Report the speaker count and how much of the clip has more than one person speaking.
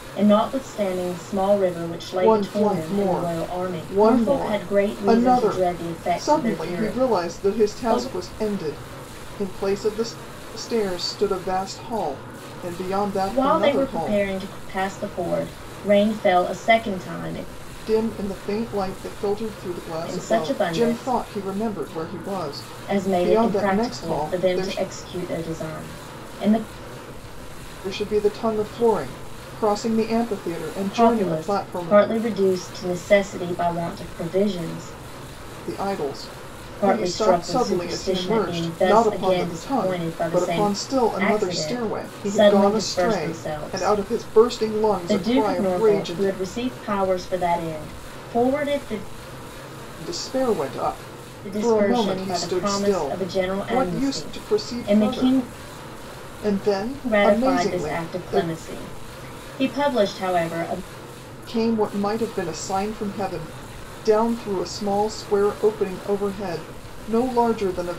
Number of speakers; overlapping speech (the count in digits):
2, about 36%